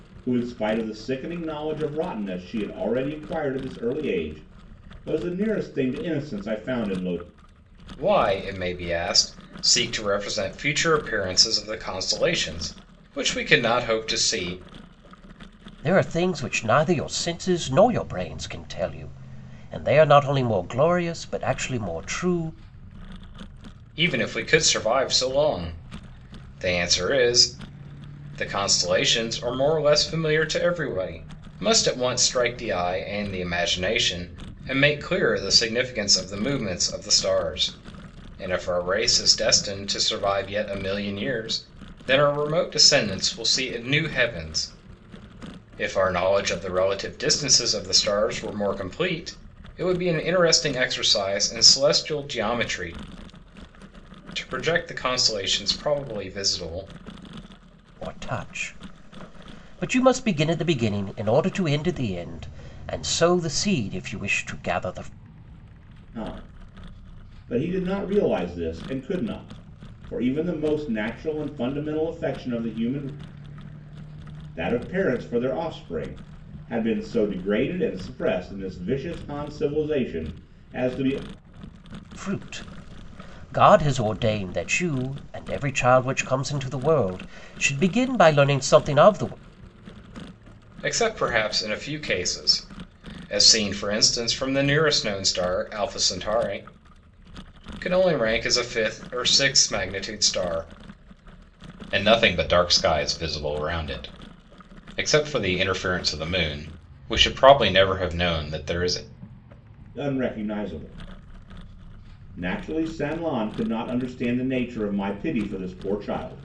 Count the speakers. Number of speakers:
3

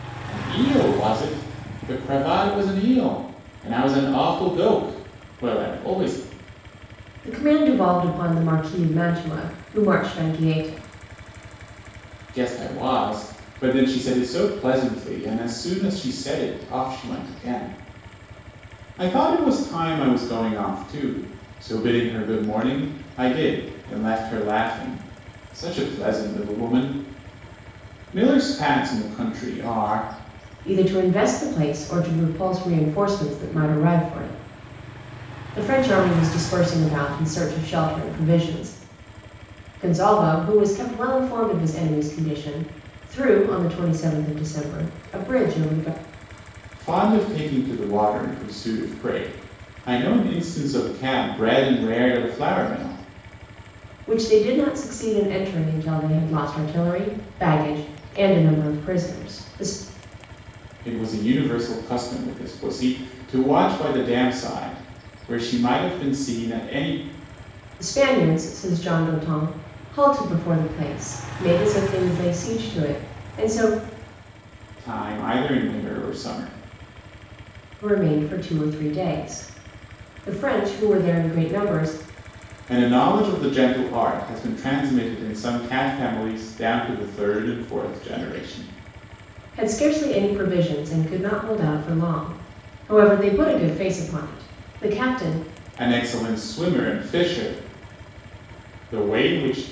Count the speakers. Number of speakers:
2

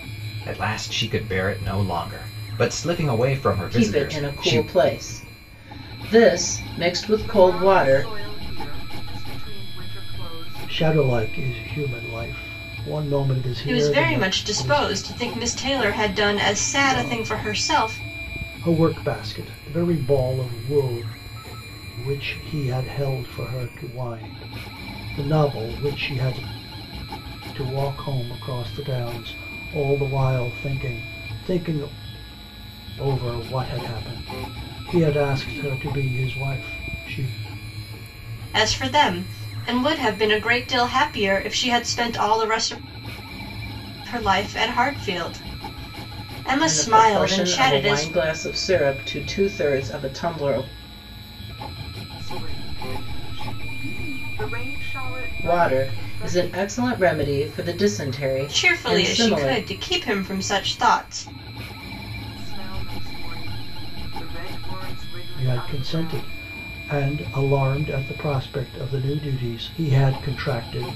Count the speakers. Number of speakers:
5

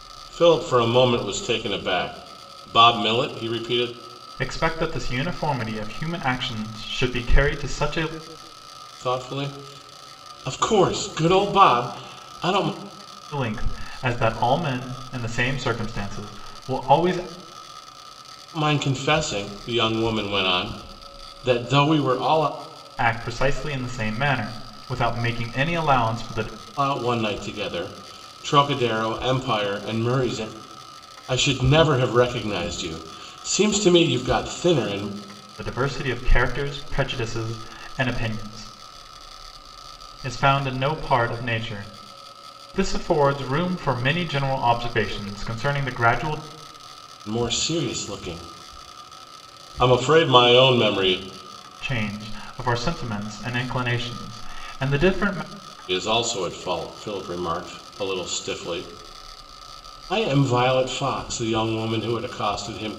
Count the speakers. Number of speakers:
2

